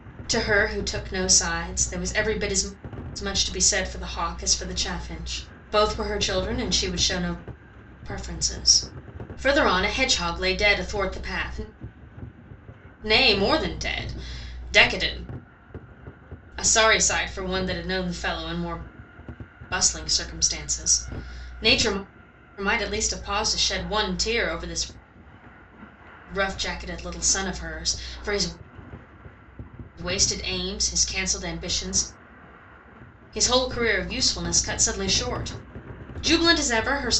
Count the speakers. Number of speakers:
1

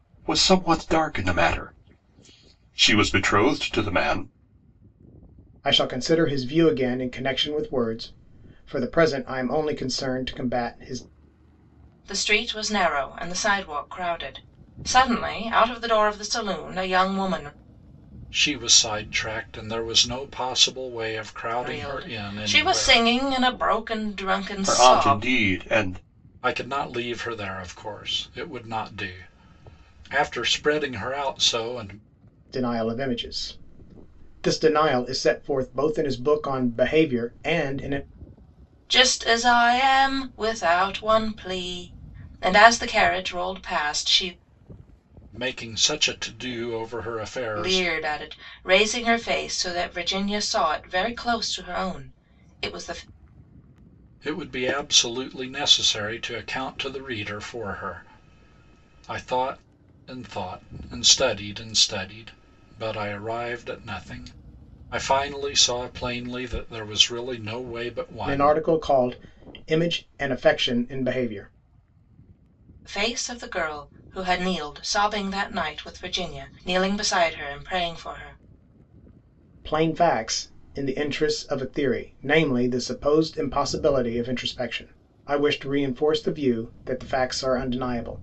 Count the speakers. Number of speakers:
4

